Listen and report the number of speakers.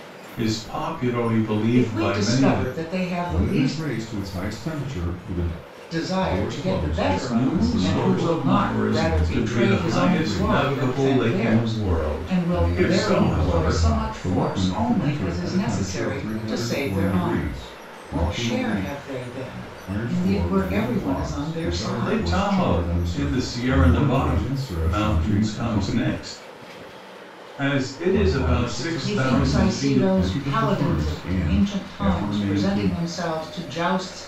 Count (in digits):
3